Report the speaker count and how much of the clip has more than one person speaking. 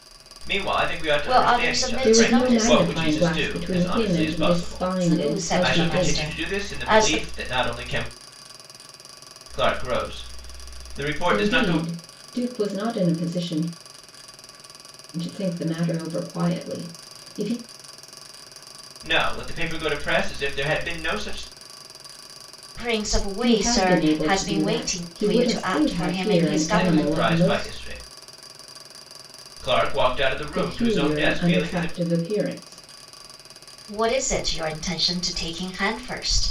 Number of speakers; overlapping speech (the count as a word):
three, about 34%